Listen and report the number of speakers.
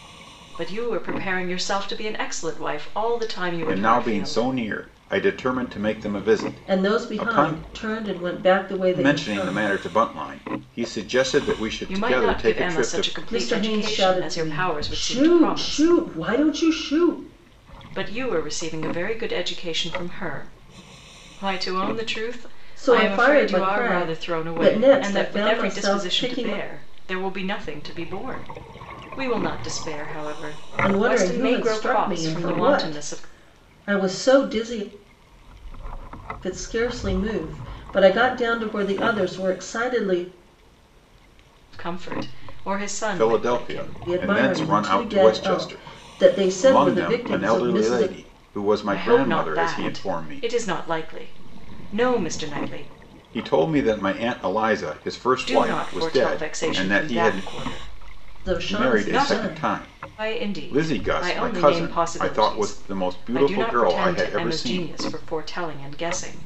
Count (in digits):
3